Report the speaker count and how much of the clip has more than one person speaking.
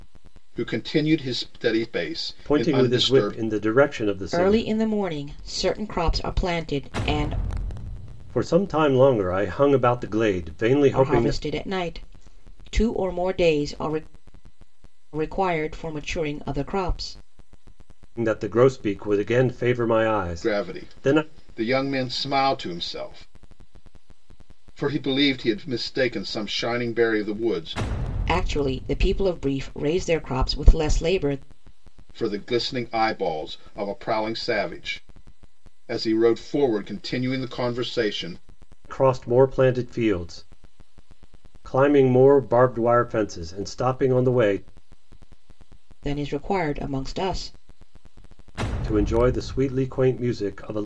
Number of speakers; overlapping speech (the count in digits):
3, about 6%